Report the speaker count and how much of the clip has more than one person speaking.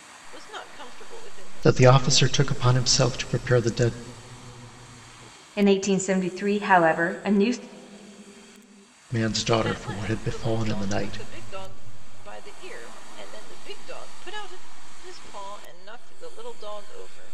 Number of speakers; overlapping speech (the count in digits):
3, about 14%